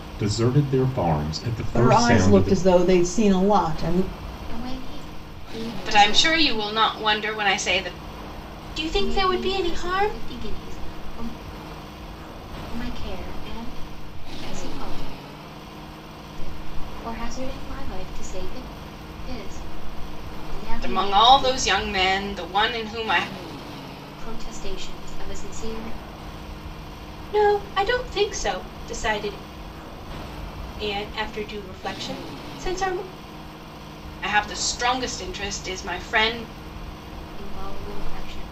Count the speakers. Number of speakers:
five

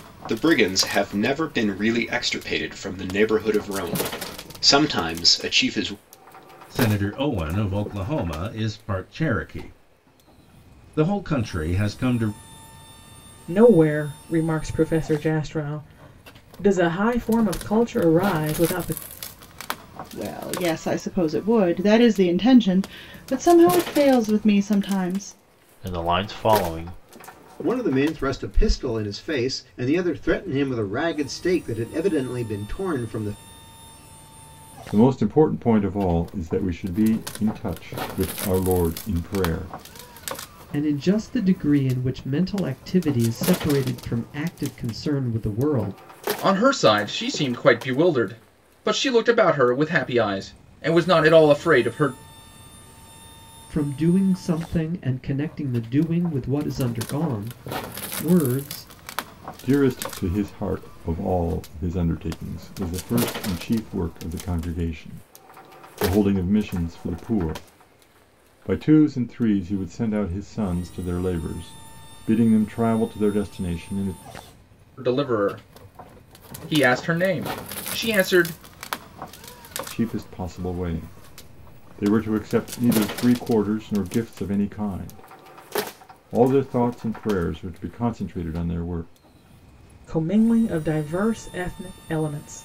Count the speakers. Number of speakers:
nine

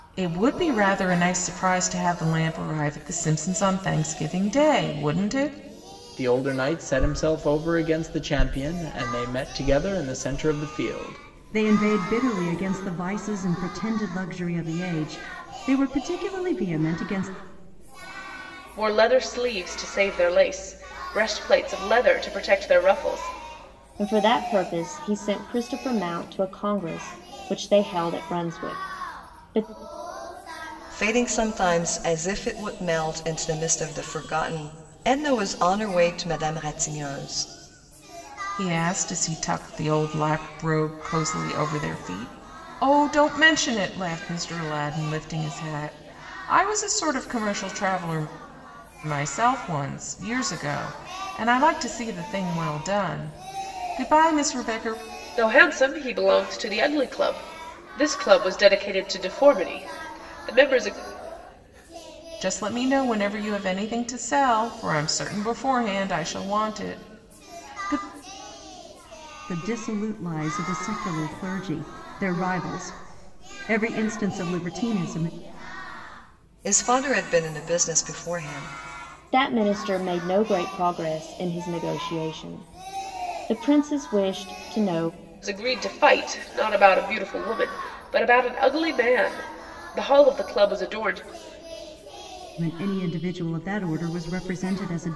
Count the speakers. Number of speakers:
six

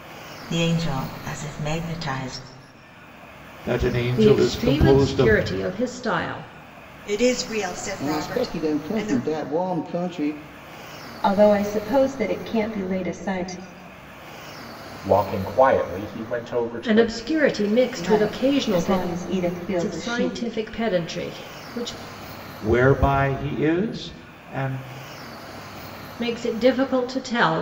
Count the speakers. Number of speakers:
seven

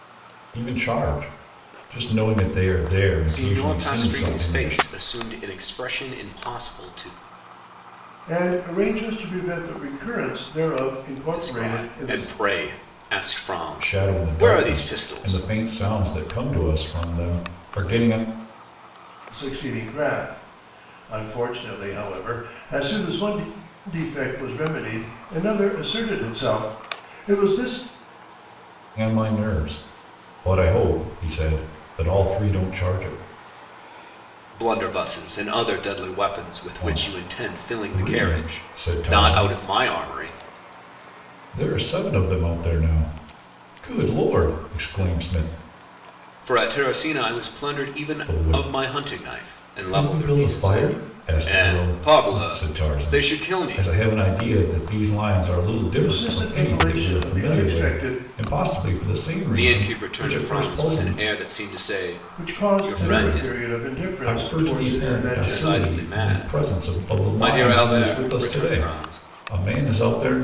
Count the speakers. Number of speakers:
three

